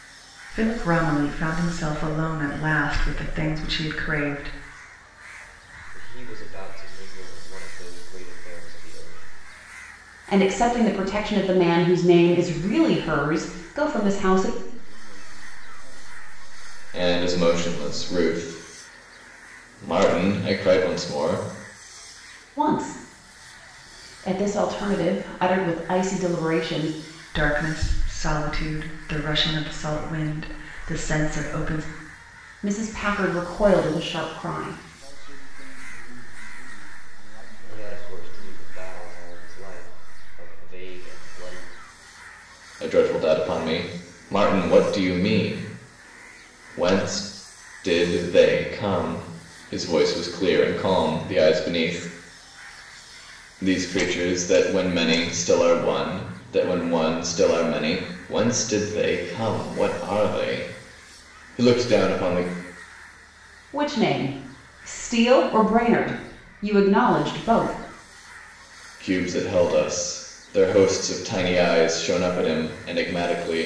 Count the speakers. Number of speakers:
5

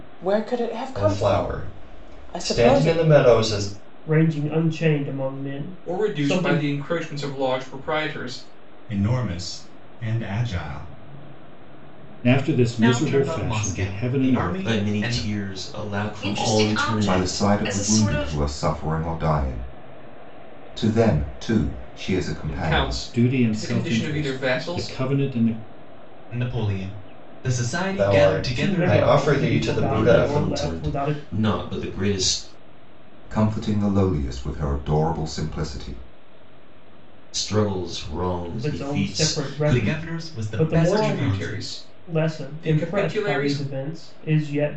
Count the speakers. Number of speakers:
10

